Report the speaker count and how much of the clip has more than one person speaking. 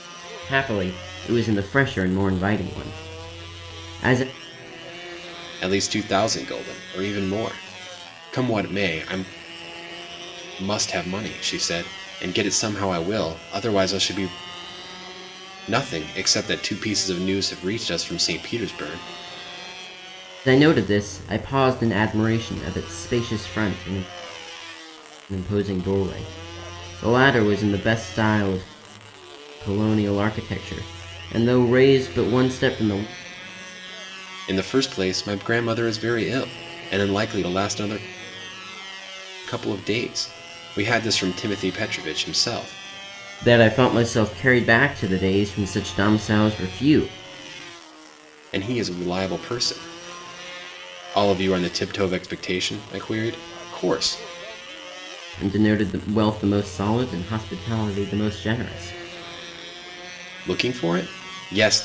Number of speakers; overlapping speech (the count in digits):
2, no overlap